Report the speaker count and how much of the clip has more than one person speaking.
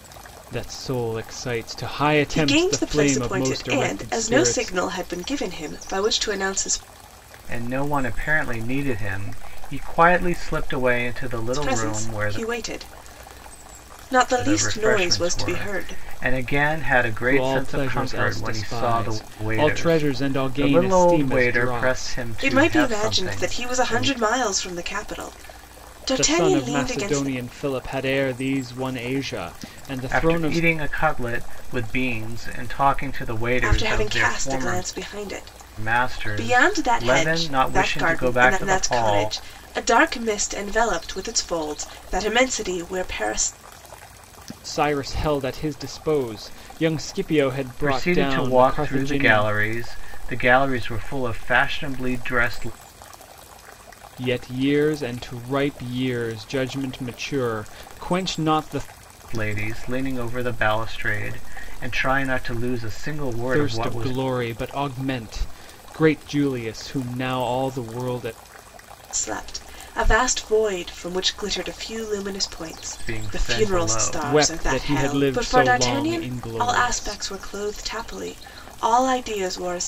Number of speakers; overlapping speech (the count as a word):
three, about 31%